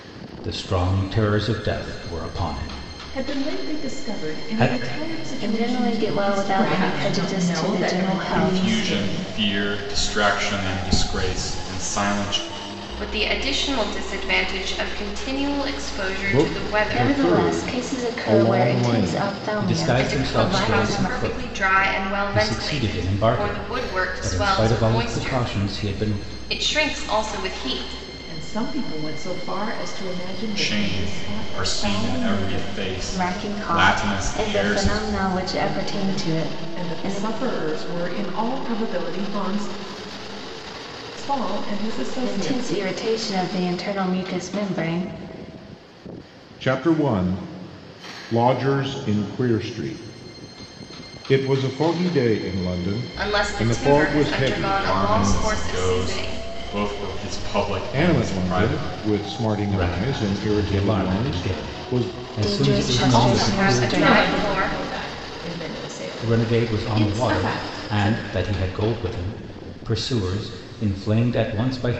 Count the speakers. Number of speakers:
7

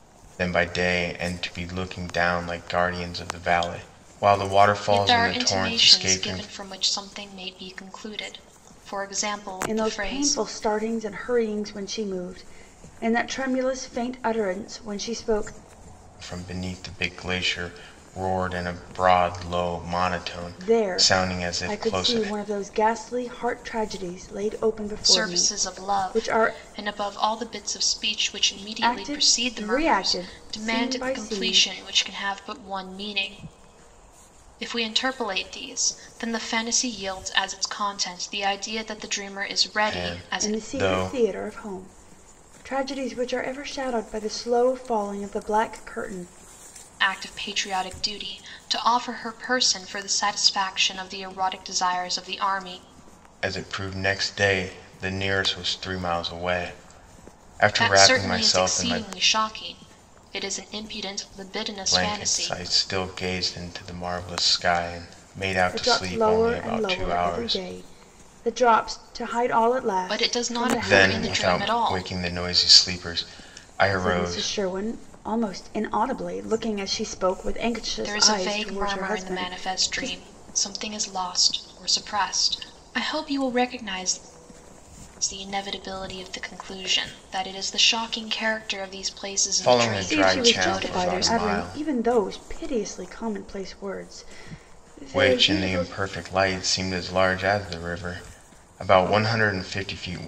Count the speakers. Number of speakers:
3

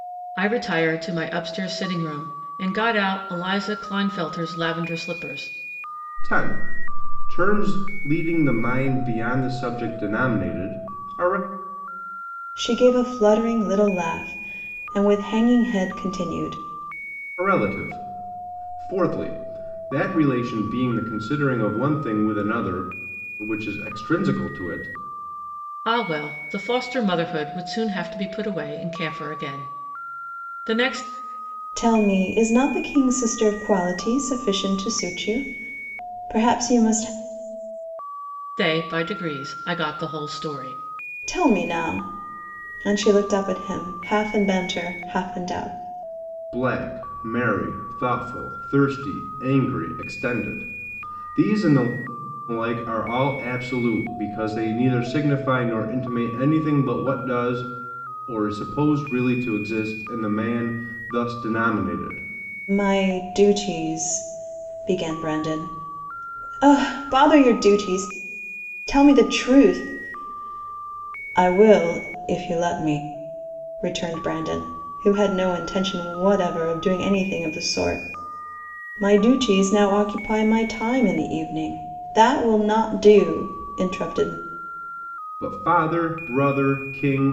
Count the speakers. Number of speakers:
3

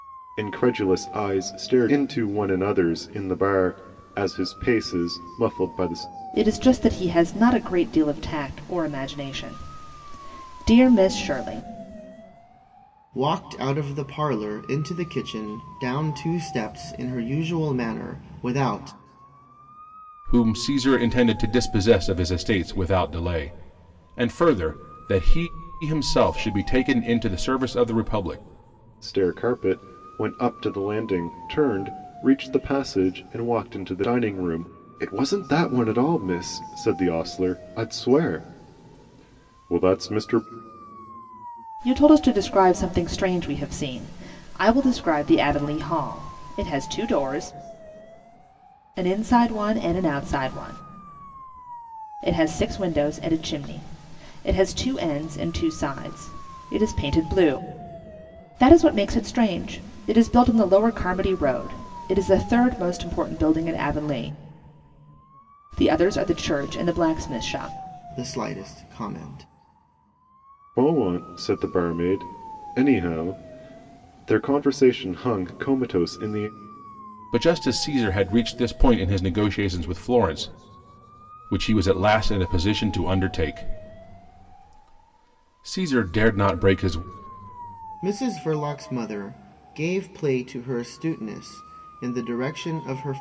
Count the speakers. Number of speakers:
4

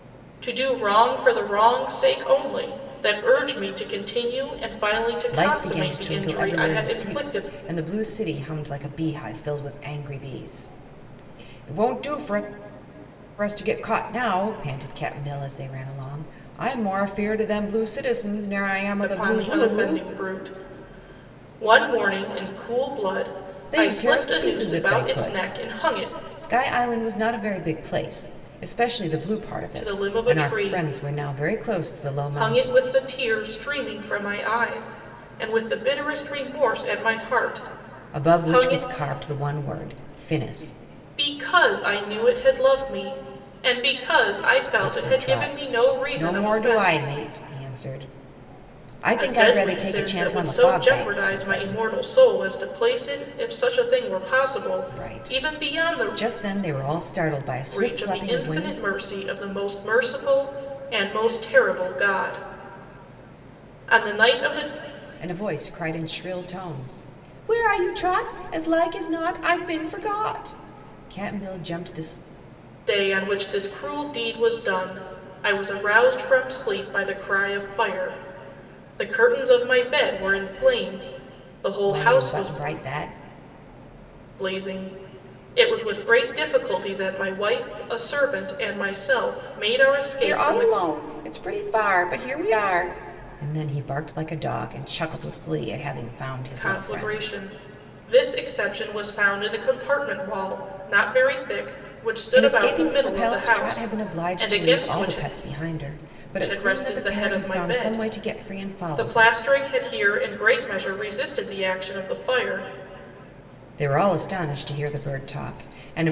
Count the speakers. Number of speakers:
2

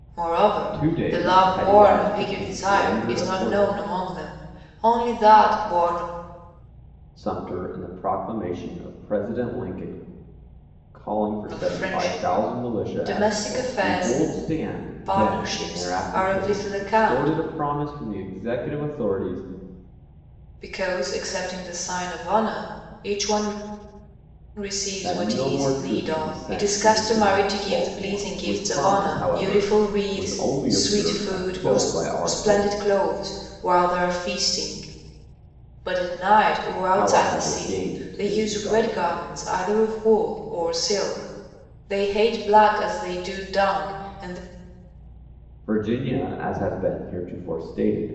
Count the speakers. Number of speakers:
2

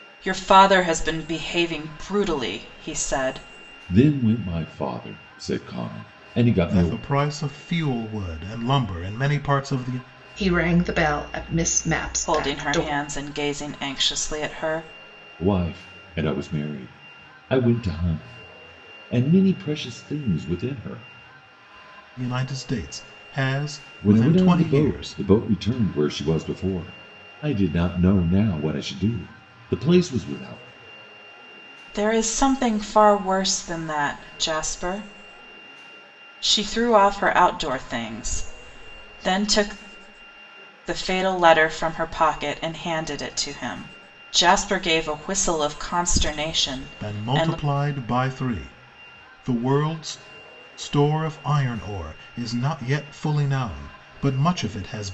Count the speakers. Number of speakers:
4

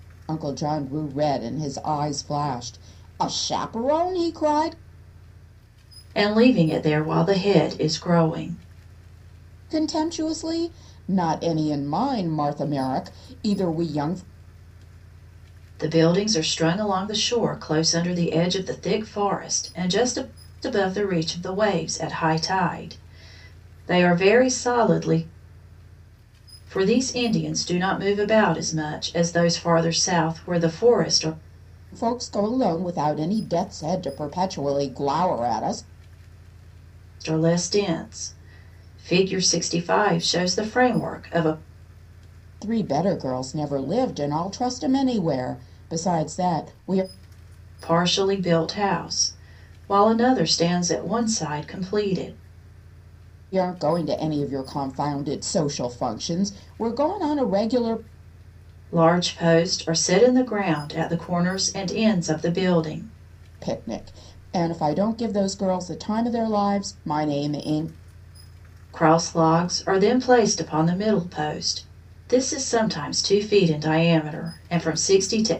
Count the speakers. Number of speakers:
2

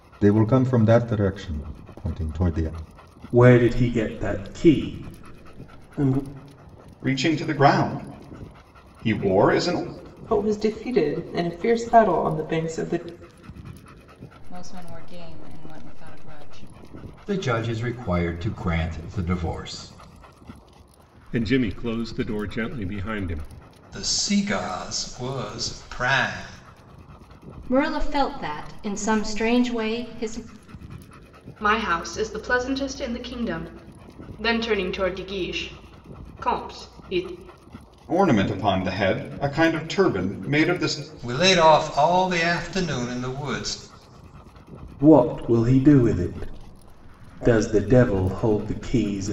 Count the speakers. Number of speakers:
10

